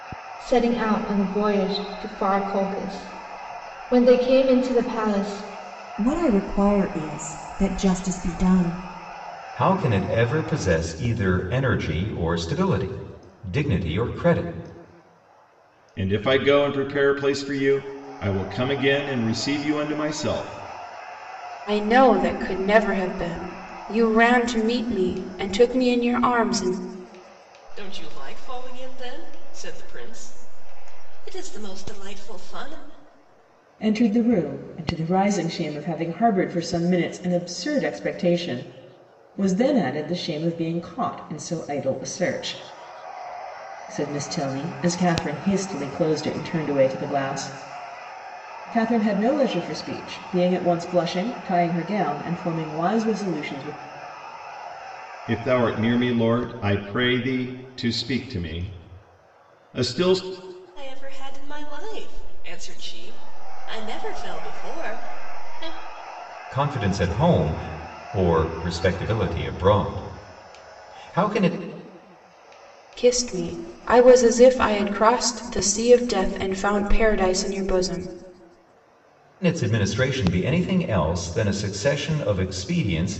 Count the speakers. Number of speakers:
seven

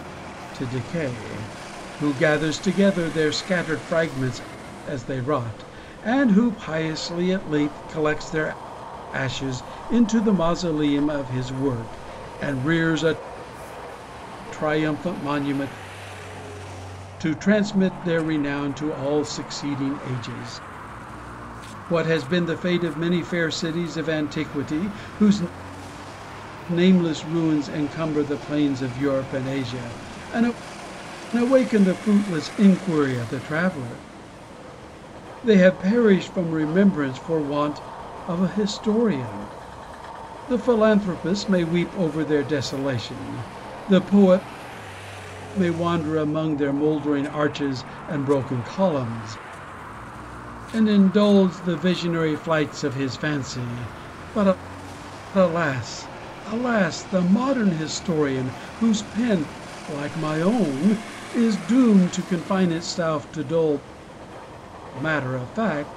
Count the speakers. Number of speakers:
one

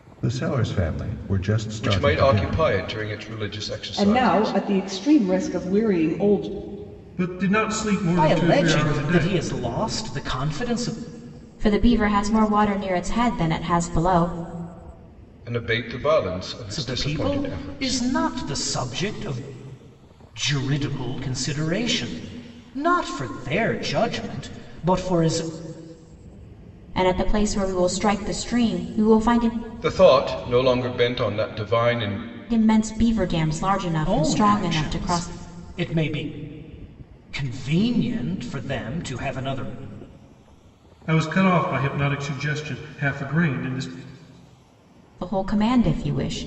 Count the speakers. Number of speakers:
six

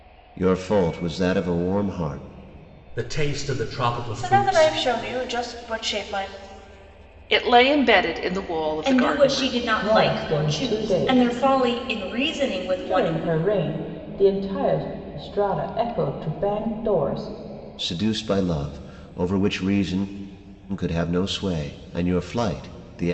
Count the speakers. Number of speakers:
six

